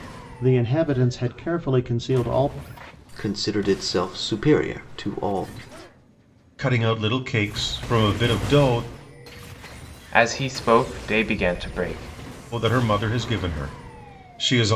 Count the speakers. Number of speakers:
4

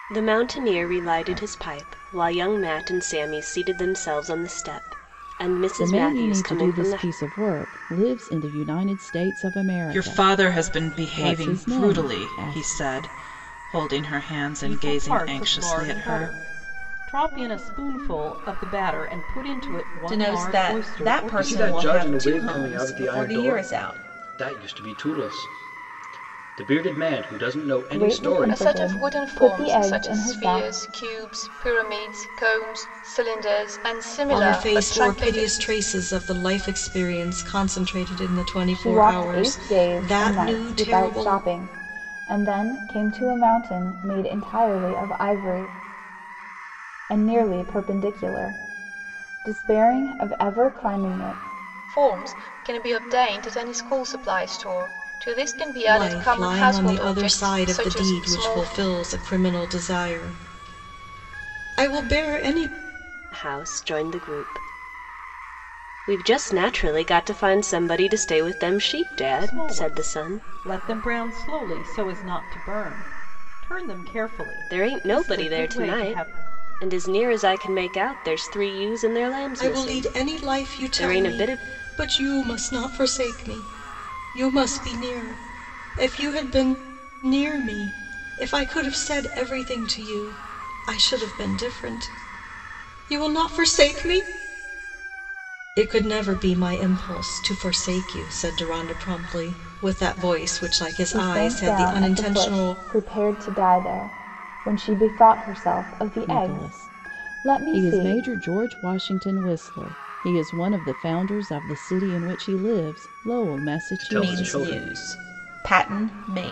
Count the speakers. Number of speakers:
9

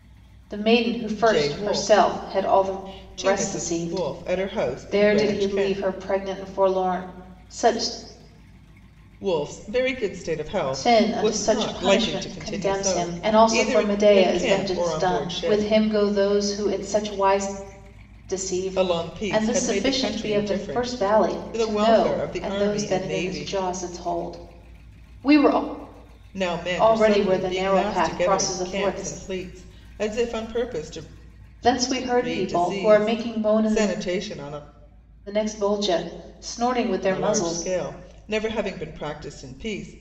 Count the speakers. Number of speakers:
2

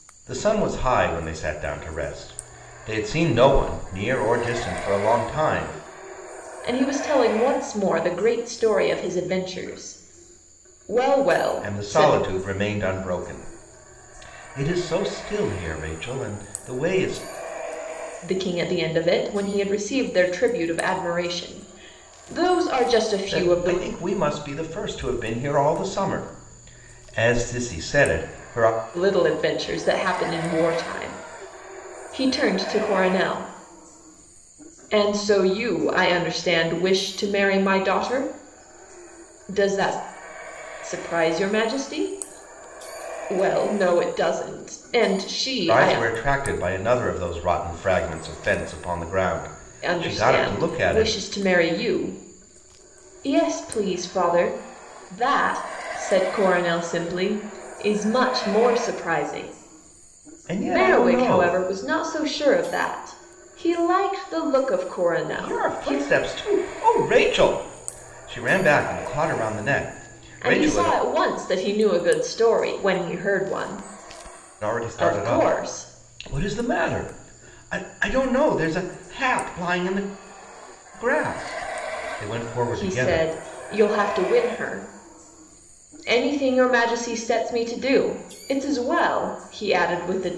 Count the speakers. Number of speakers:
2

